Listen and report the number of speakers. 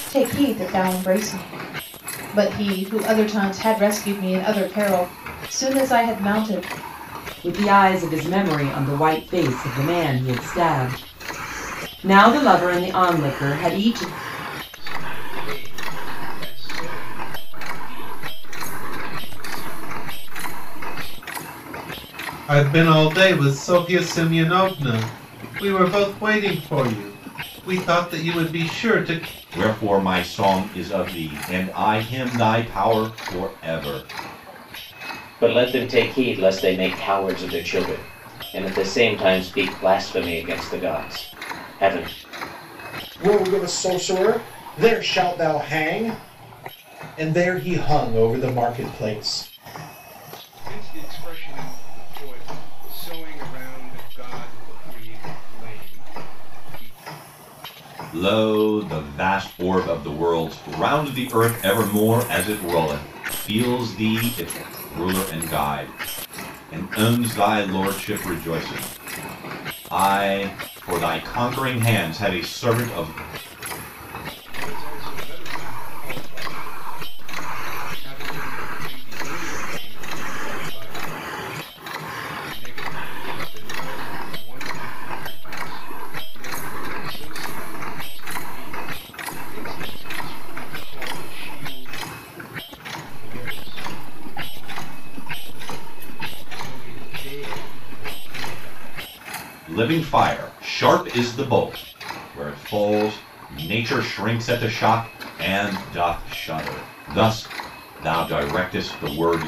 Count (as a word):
seven